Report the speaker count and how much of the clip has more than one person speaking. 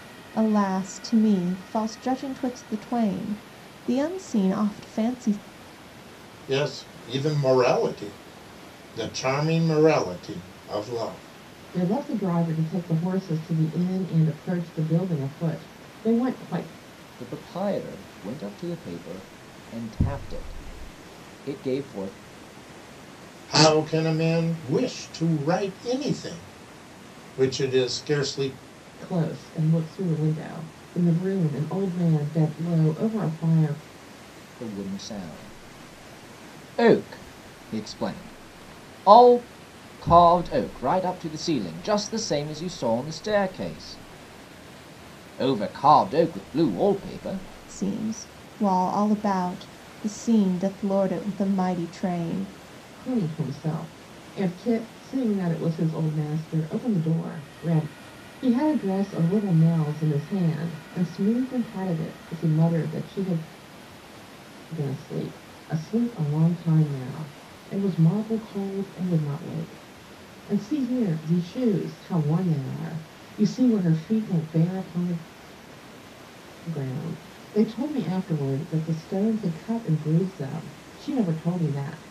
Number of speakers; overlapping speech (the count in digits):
4, no overlap